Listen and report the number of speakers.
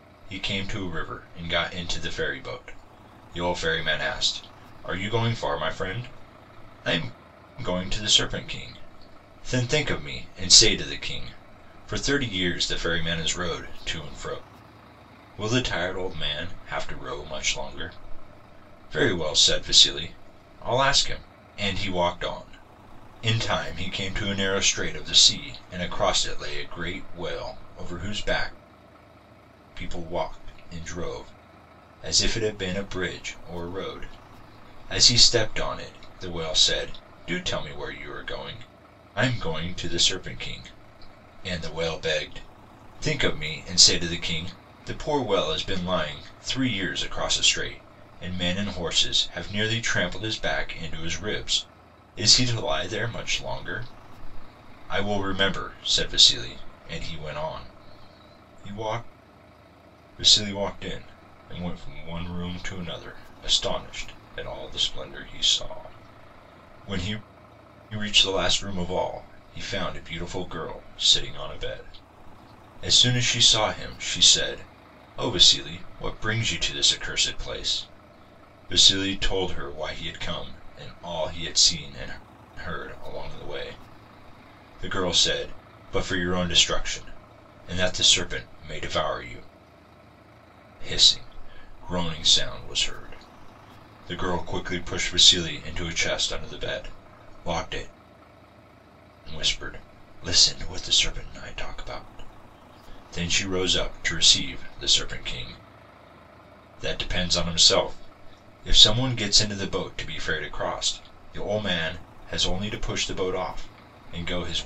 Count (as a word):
one